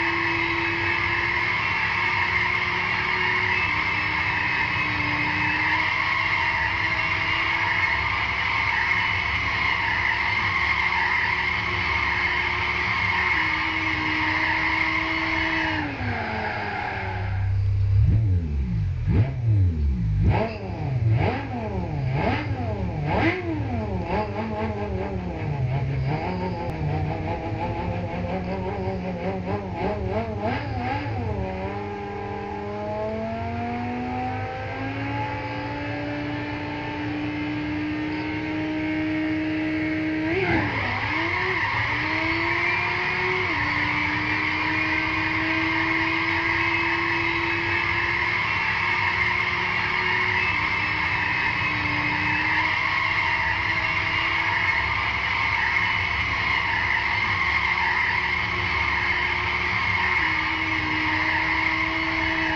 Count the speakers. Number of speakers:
0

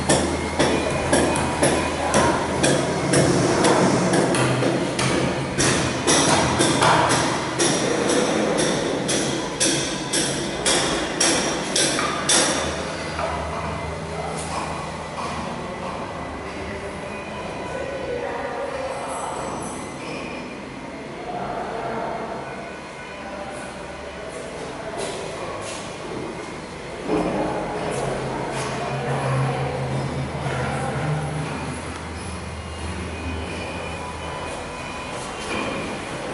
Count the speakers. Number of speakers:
0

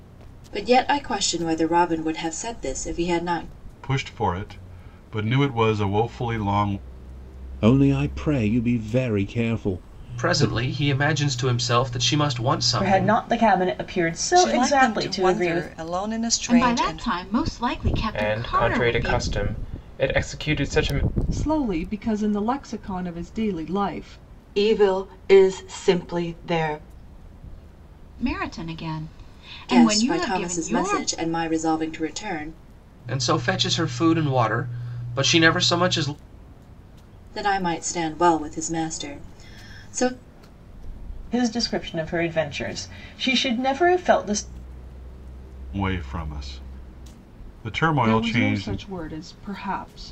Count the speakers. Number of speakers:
10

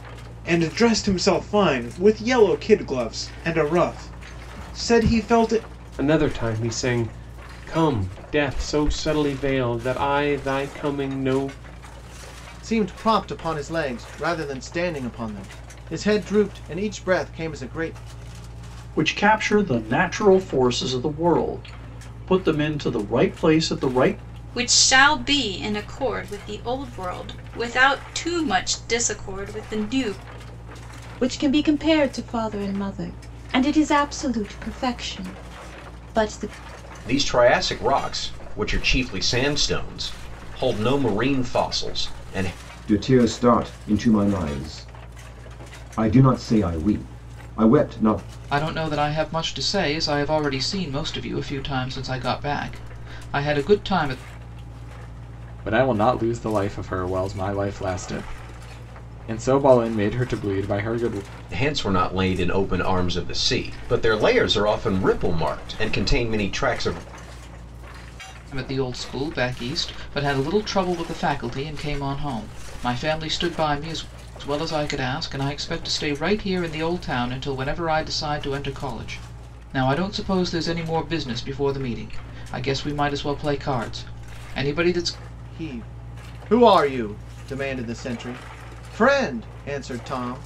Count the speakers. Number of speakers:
10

